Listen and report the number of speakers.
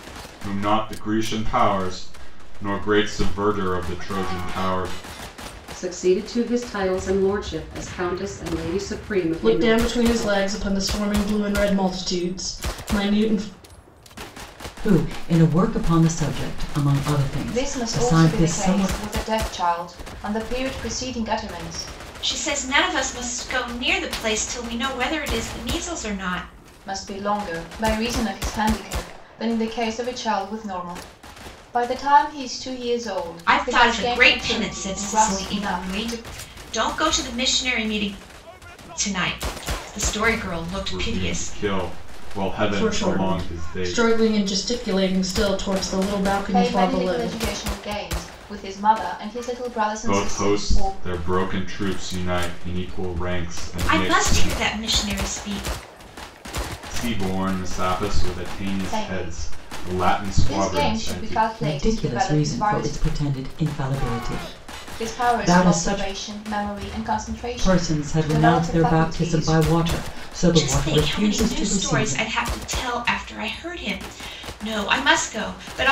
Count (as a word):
six